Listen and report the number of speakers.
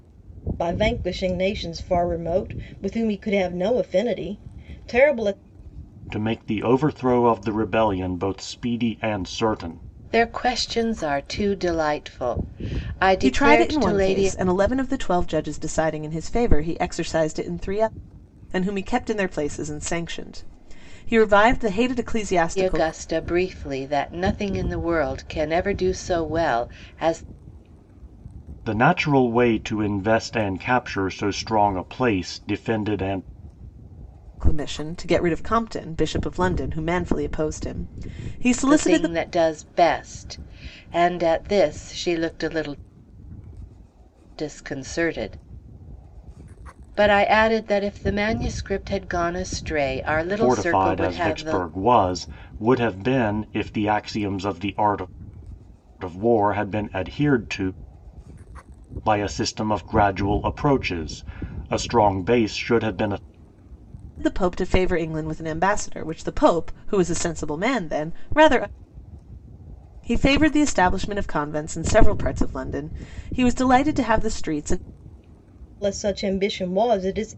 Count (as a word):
four